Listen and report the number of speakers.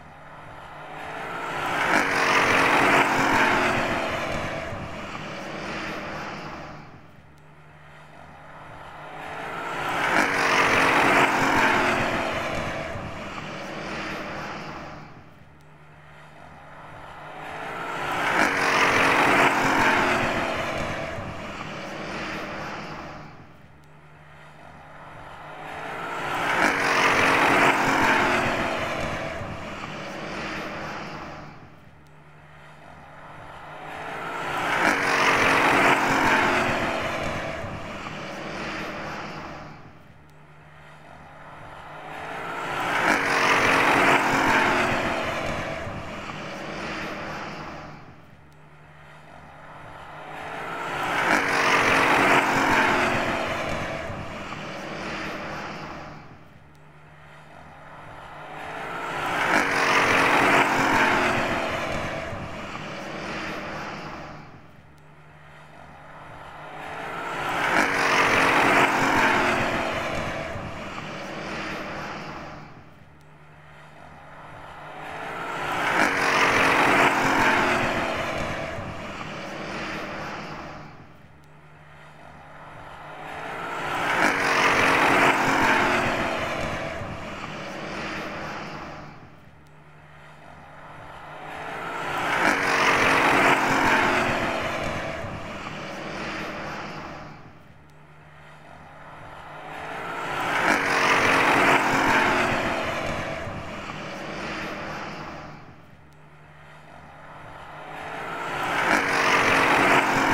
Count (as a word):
zero